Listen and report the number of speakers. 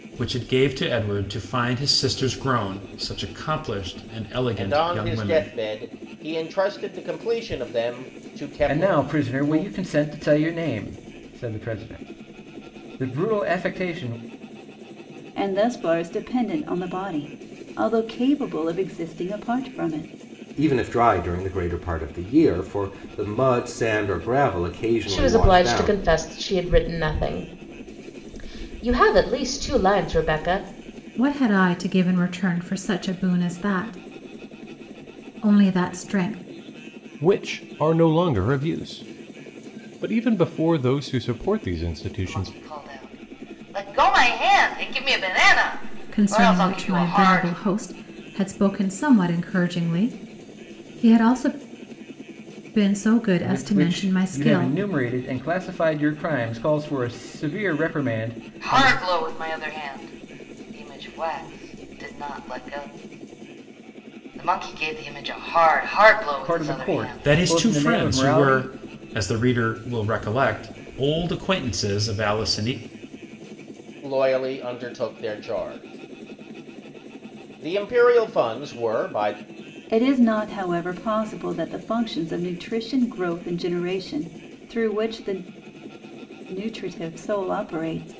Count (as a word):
nine